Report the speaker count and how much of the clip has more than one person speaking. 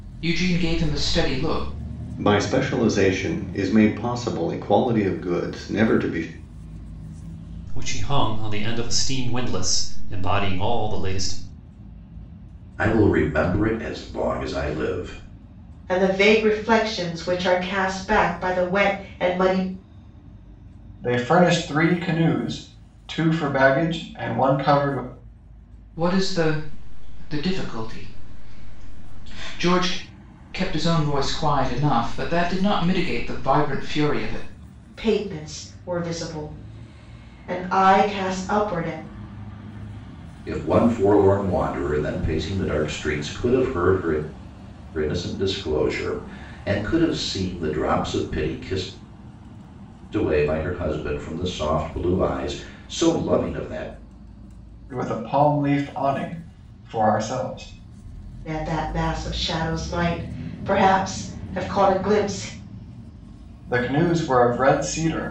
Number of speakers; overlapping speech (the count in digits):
6, no overlap